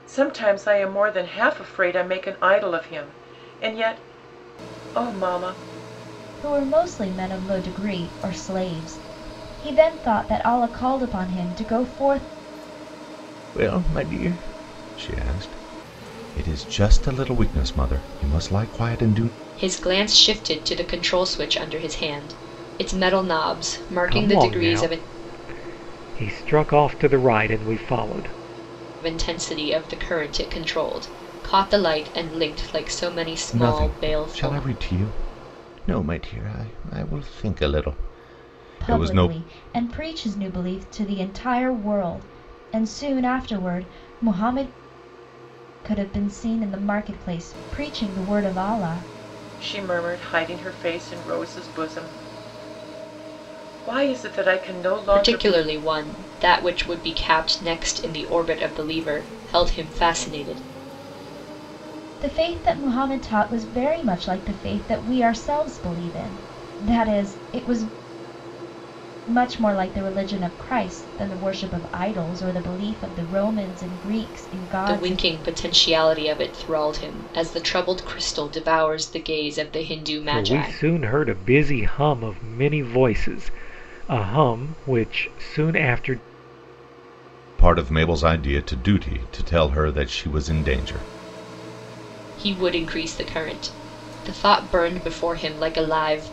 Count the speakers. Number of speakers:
5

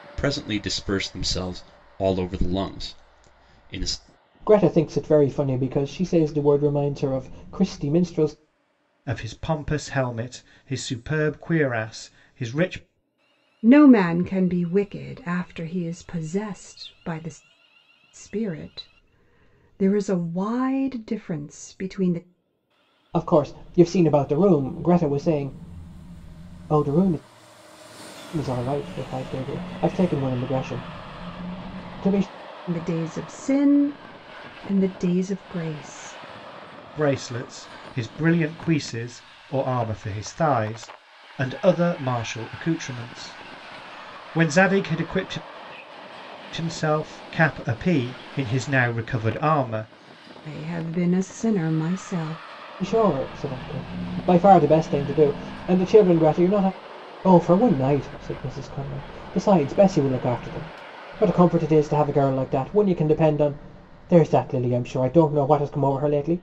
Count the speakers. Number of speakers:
4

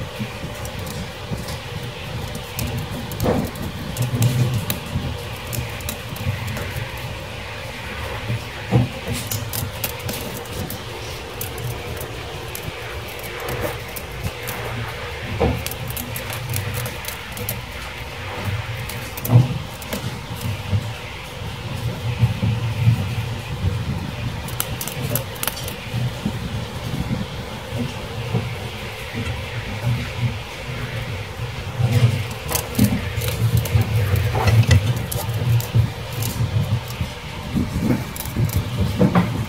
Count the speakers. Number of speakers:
0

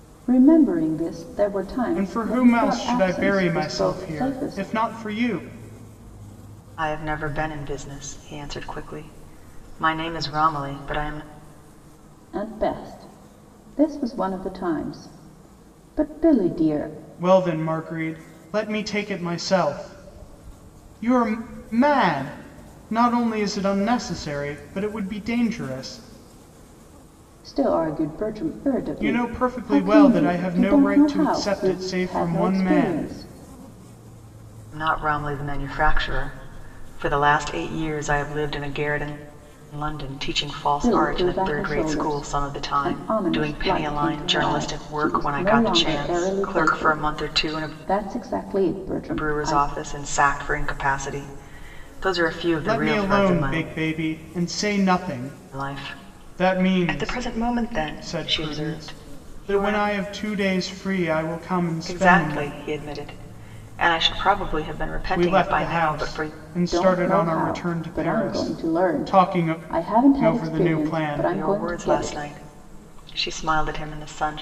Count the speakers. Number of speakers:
3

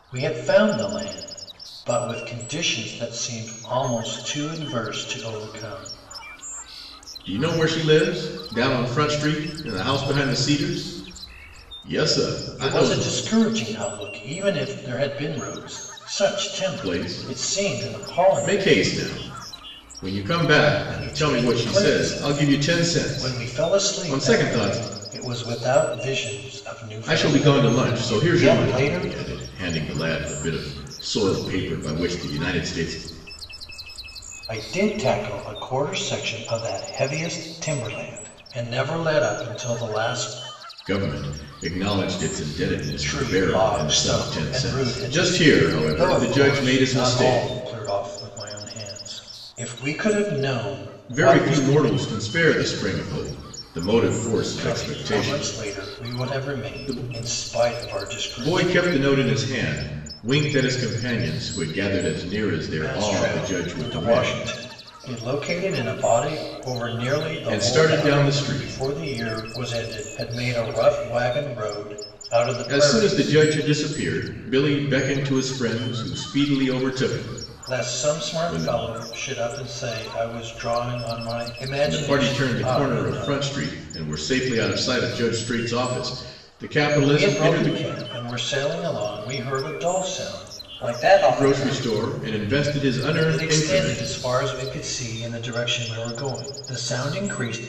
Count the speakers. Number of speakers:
2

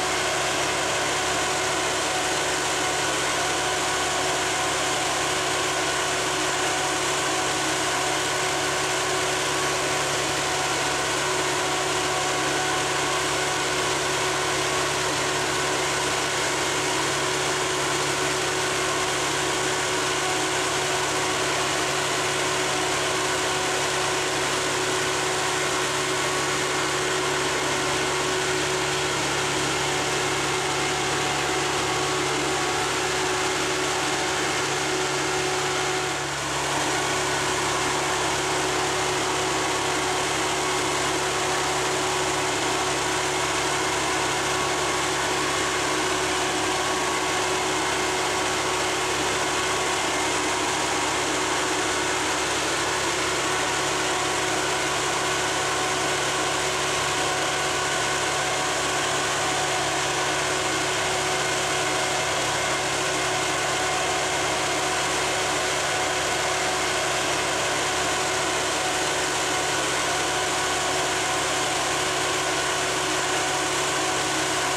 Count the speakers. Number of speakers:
0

